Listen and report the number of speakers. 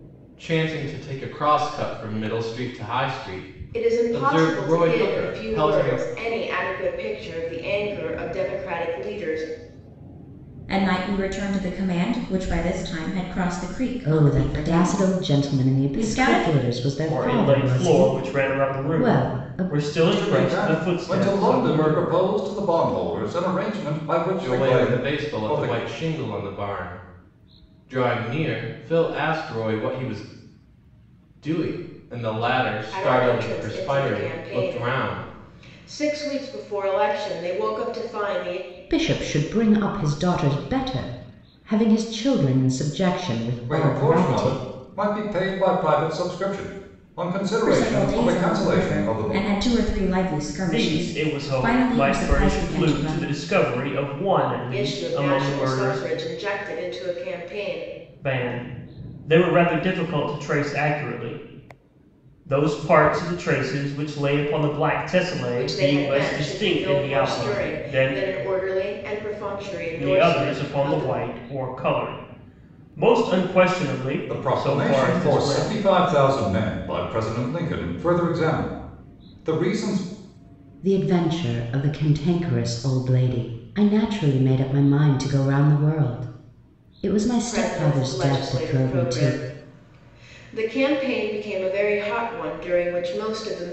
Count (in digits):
6